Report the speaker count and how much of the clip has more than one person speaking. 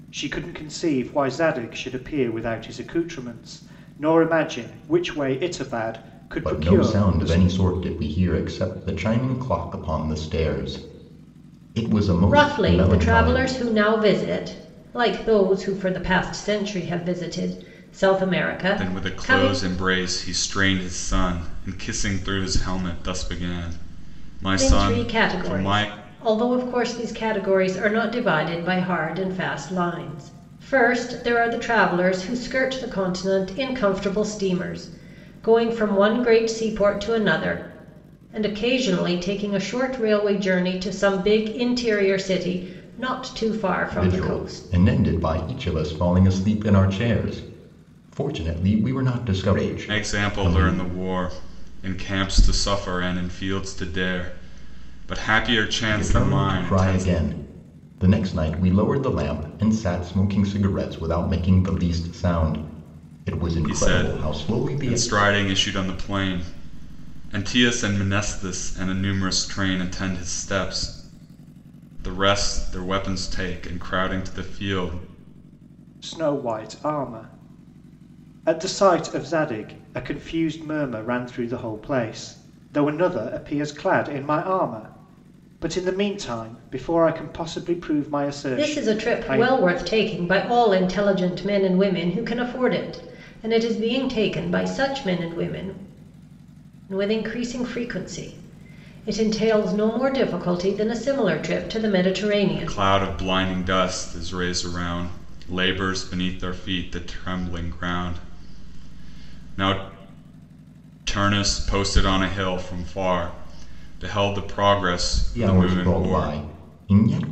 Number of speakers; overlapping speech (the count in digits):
4, about 9%